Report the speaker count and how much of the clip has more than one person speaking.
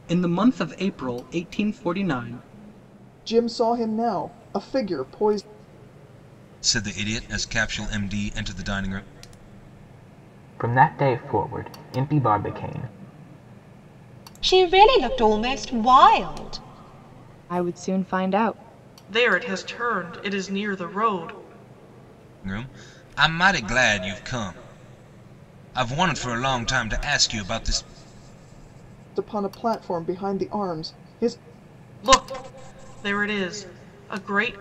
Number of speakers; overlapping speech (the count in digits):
7, no overlap